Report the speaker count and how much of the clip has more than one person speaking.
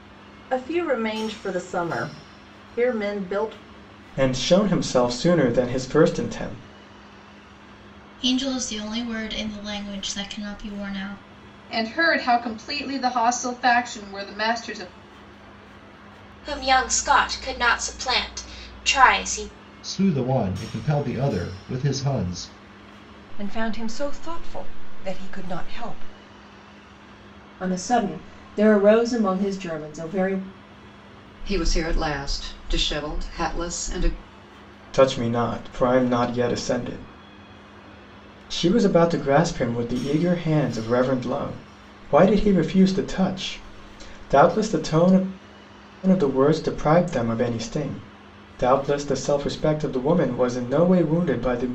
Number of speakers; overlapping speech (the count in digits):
9, no overlap